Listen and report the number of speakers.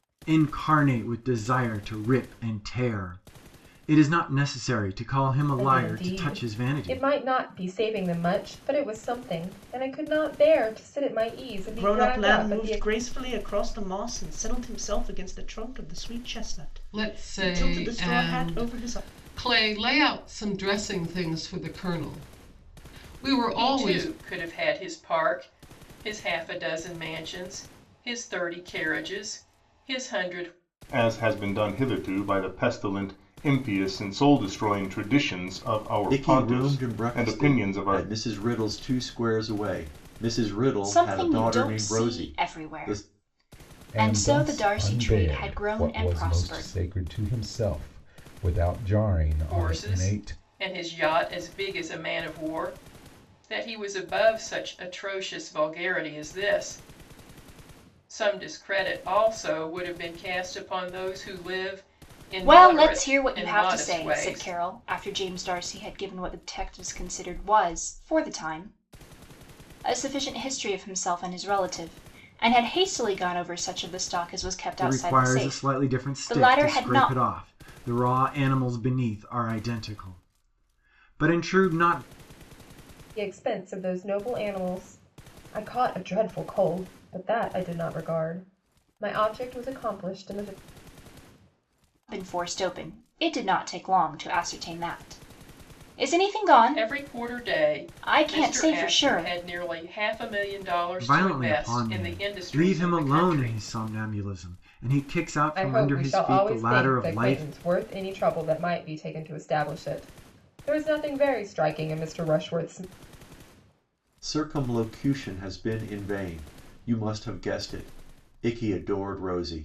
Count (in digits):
9